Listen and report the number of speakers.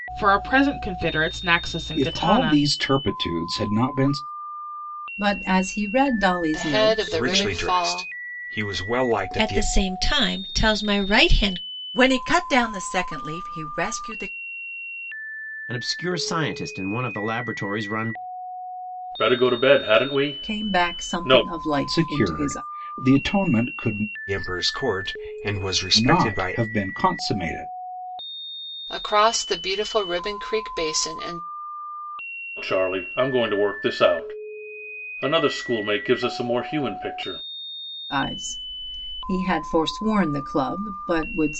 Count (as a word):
nine